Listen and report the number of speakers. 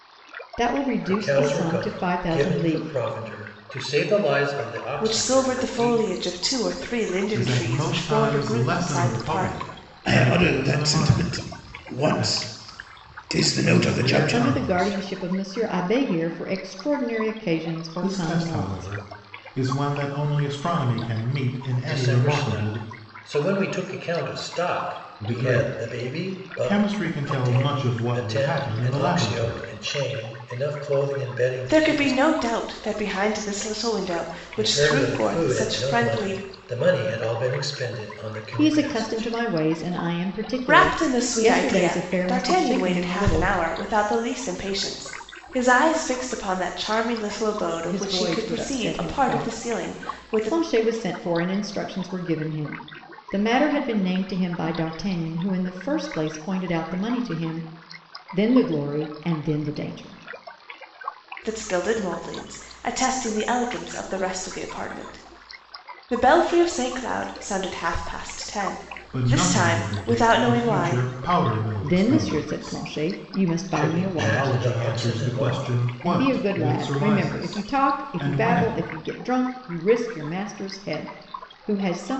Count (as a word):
five